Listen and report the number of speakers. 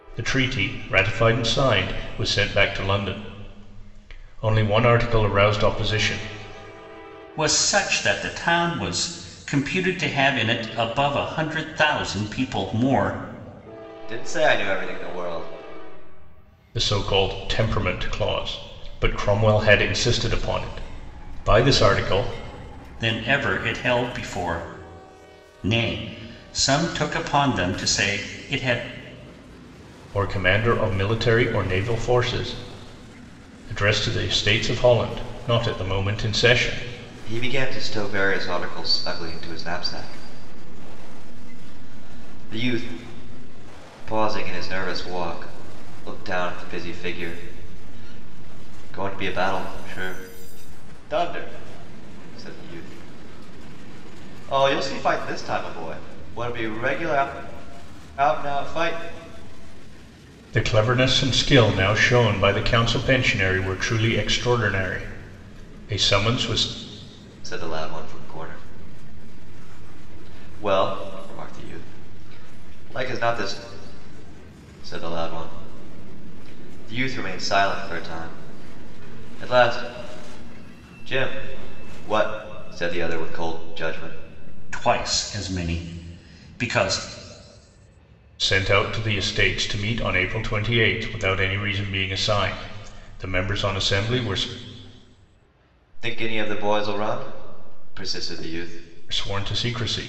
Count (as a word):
three